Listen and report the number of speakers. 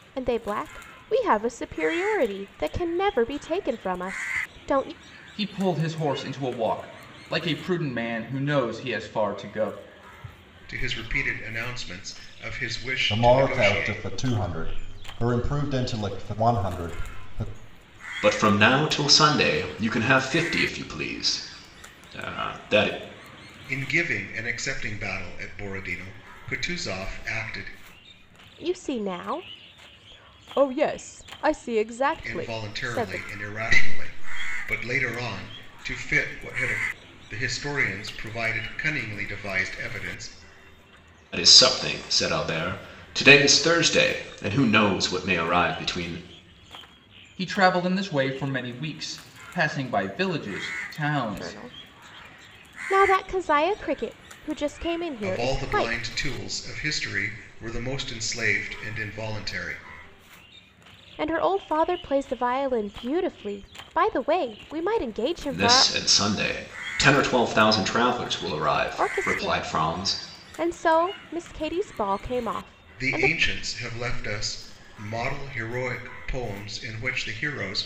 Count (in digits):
5